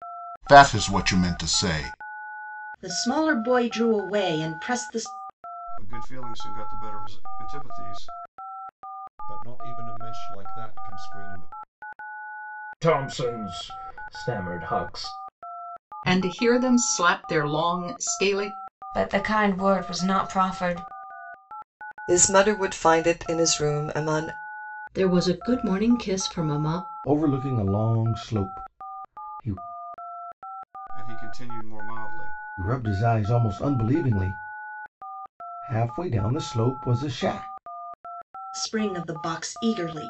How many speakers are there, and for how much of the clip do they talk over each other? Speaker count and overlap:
ten, no overlap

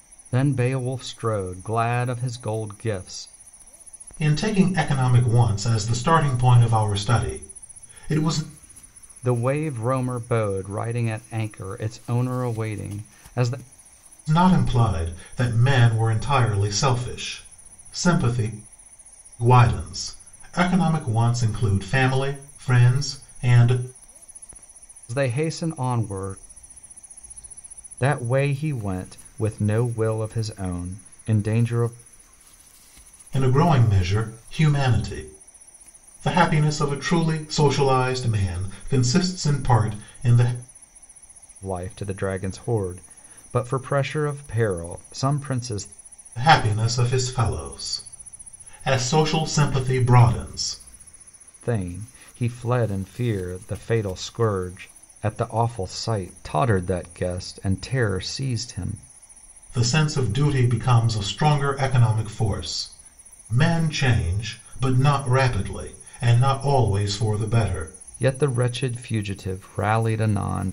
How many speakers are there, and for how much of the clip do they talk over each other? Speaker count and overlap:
two, no overlap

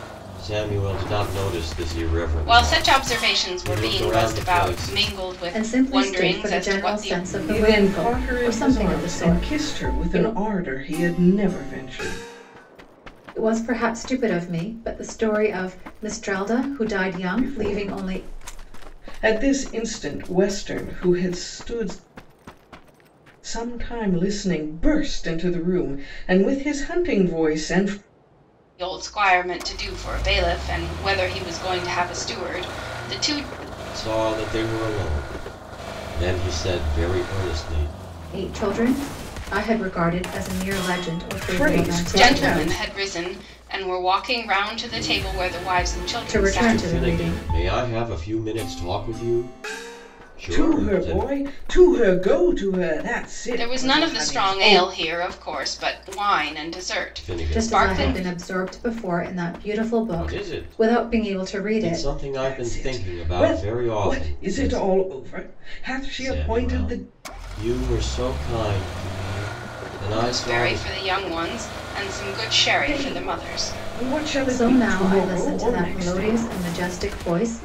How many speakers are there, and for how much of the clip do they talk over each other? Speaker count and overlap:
four, about 30%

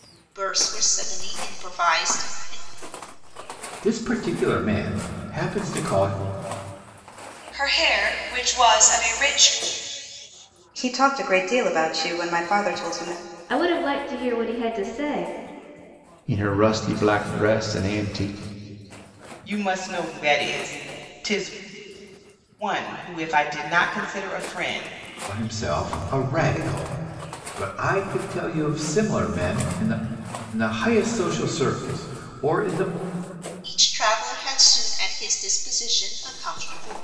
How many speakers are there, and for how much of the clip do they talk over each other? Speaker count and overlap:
seven, no overlap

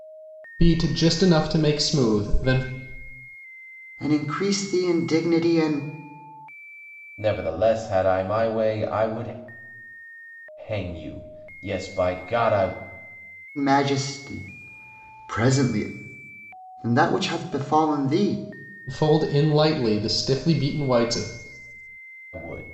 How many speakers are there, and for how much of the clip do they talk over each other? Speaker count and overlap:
three, no overlap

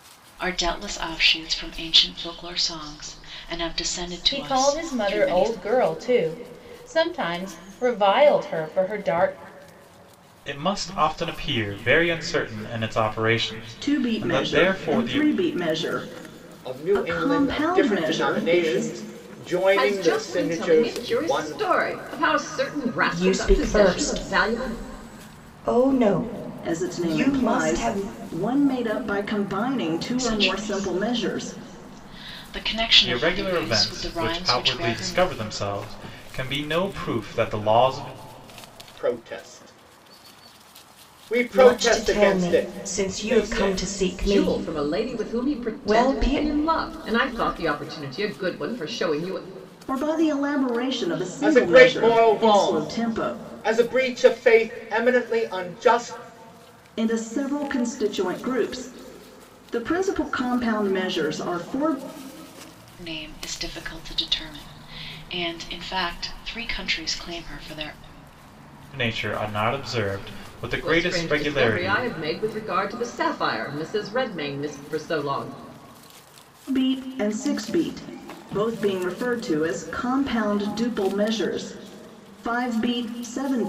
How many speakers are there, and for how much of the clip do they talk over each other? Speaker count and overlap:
seven, about 26%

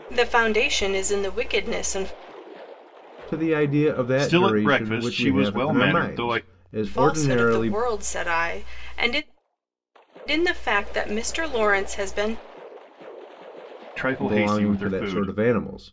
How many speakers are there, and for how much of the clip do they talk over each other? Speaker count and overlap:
three, about 27%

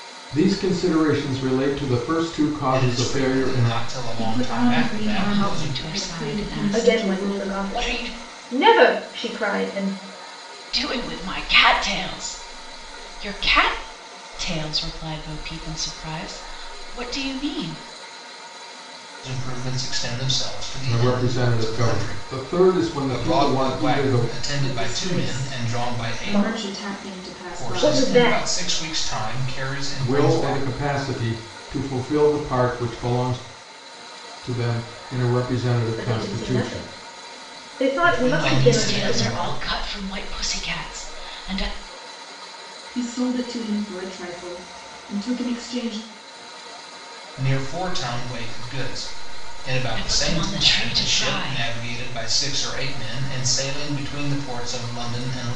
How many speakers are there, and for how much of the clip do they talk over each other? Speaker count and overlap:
five, about 30%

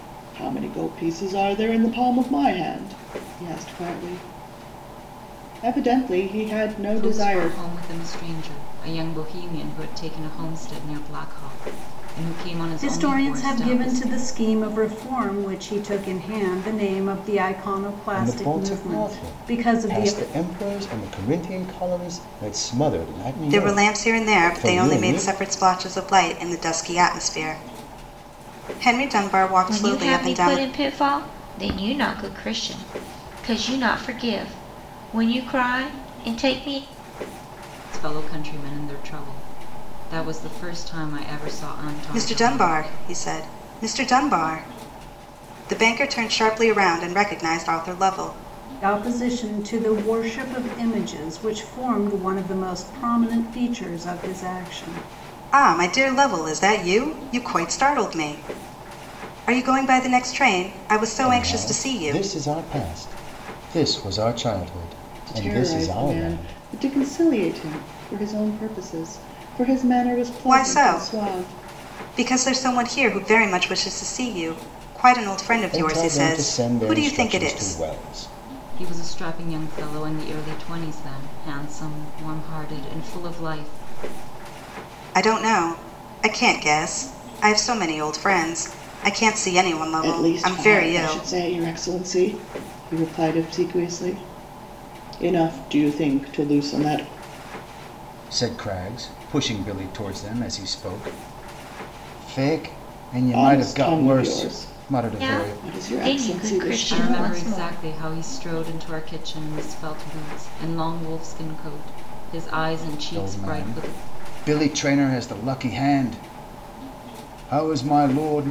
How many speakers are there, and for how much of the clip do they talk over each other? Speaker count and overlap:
six, about 17%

